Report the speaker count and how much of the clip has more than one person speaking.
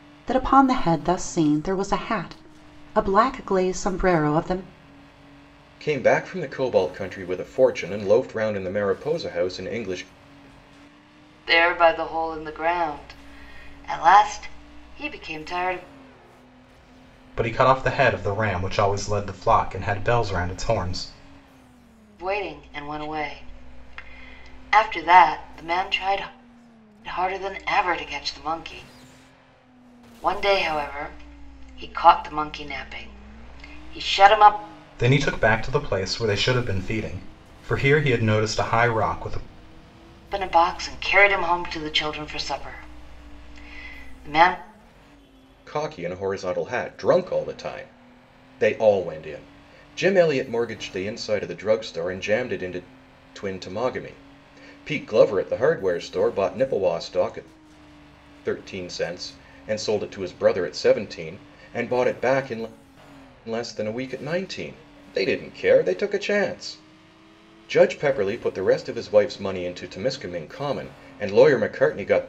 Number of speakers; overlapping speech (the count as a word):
four, no overlap